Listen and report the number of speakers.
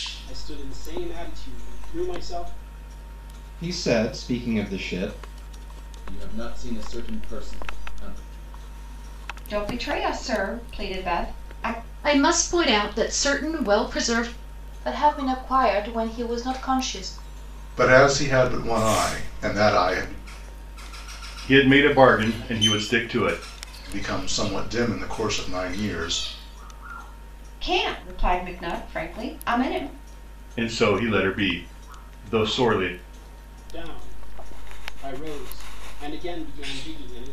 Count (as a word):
eight